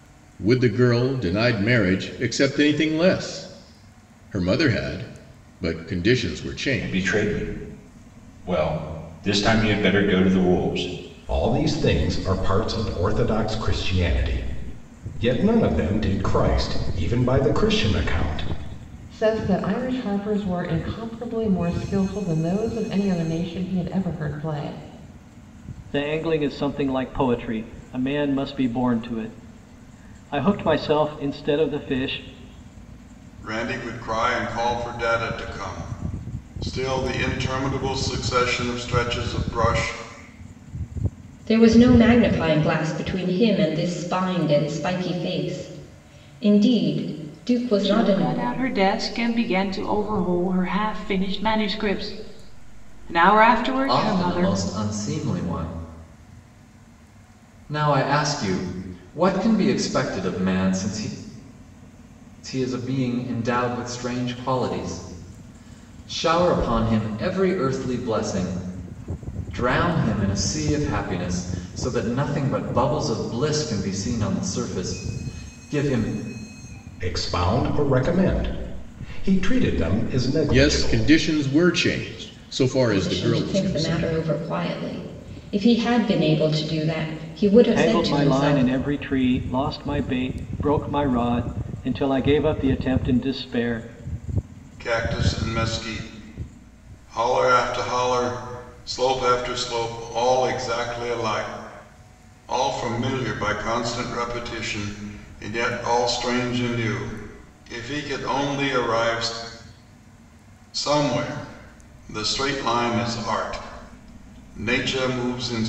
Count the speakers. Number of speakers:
9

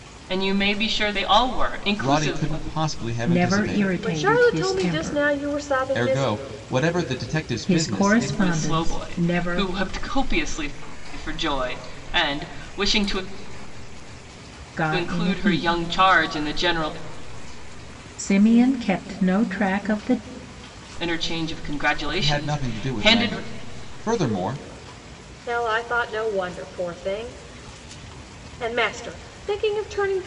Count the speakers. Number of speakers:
4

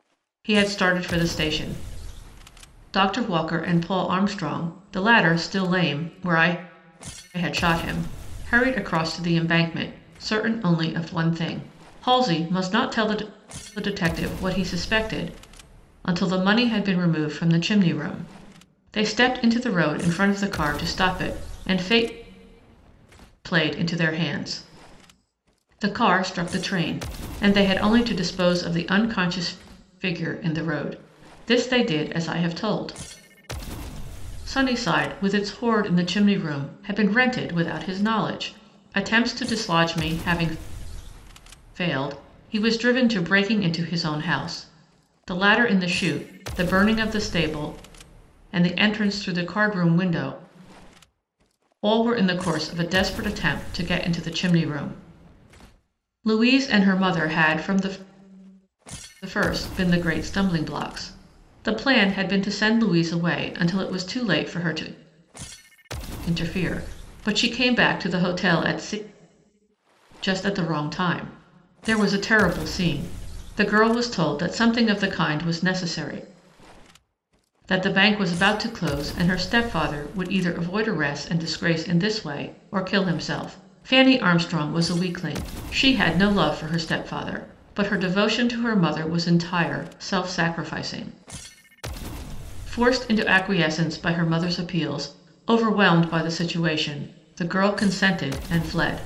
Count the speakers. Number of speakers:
1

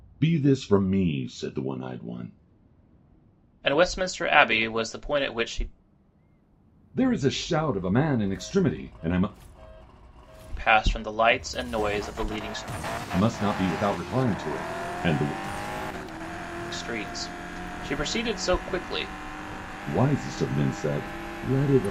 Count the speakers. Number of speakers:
2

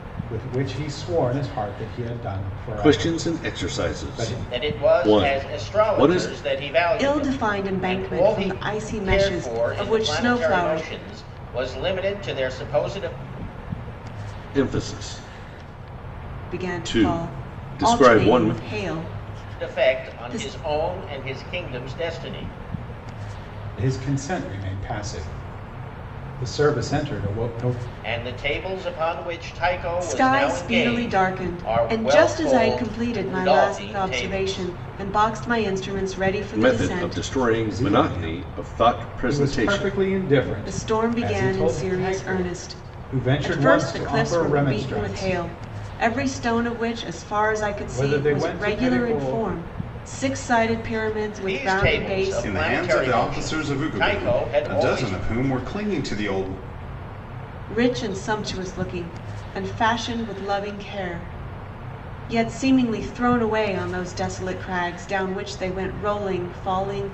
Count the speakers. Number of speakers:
4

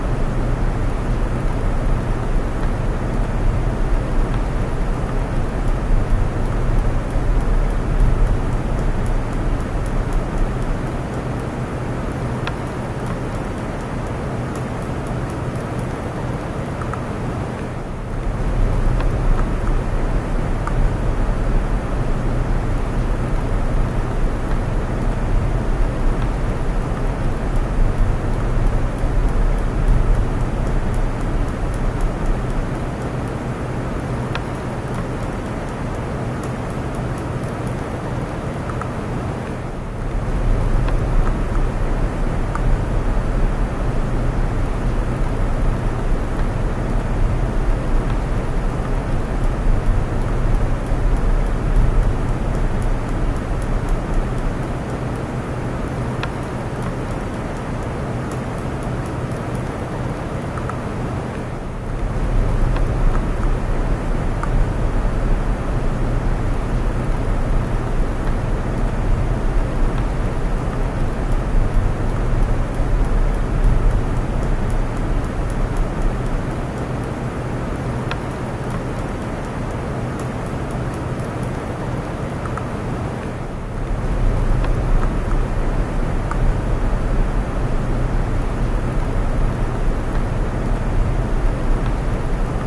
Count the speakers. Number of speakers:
0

